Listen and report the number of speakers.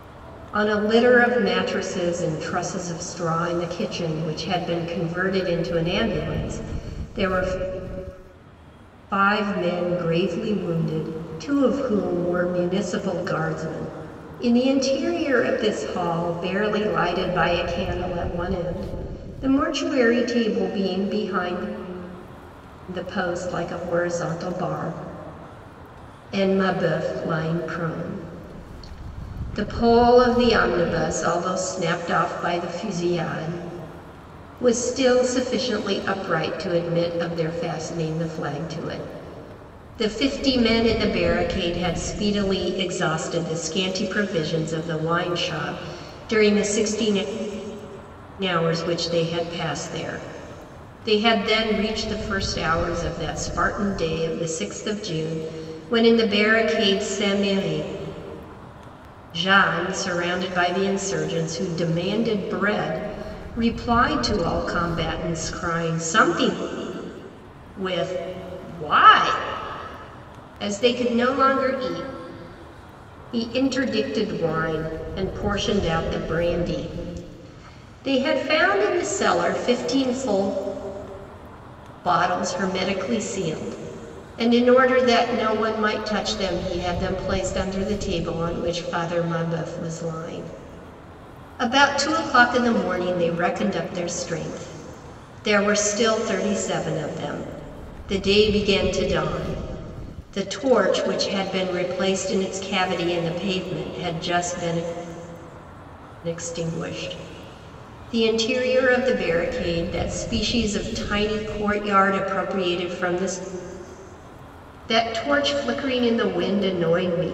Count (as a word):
one